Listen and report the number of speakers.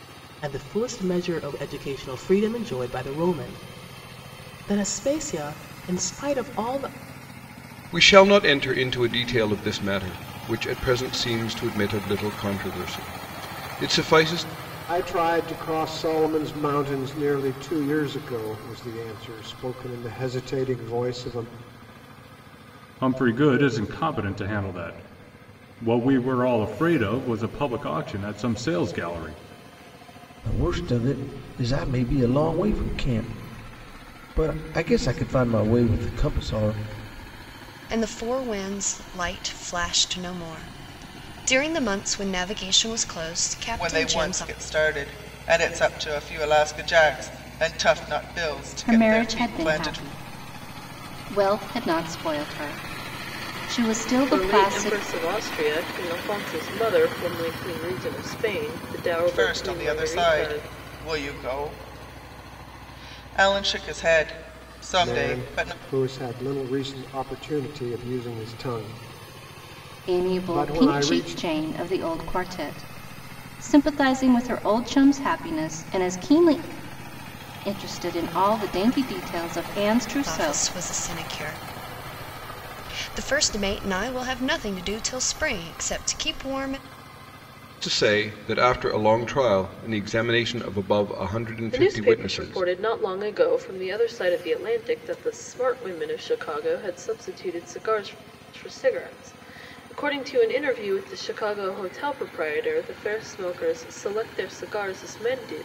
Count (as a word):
nine